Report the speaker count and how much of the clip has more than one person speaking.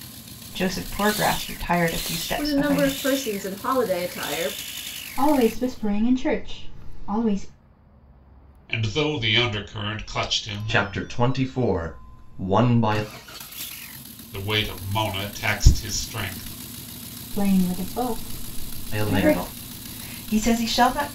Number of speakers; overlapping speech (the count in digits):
5, about 8%